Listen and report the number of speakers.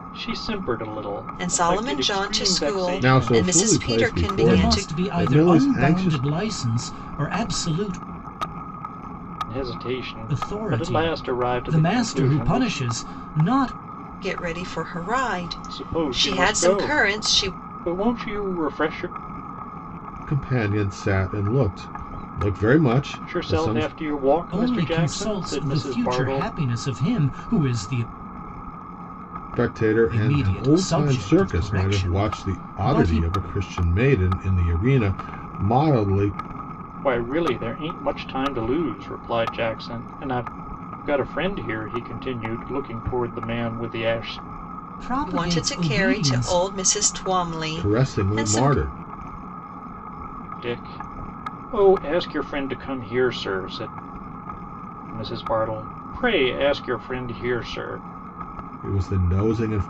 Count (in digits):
4